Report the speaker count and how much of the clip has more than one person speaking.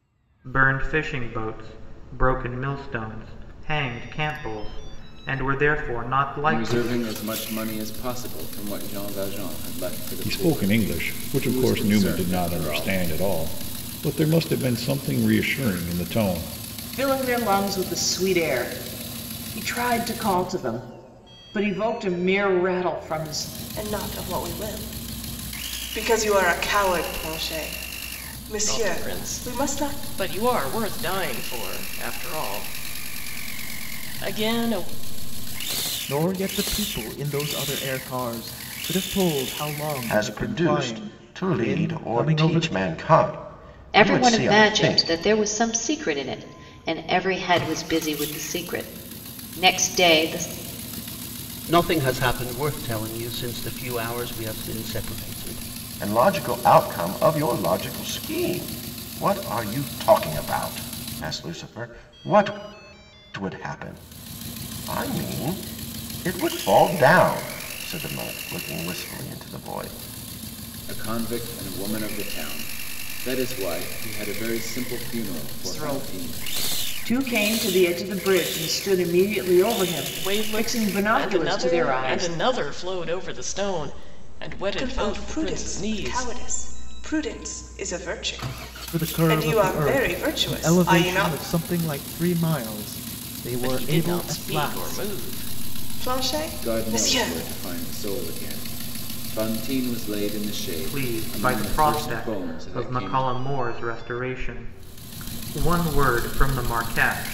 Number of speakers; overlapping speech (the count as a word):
ten, about 19%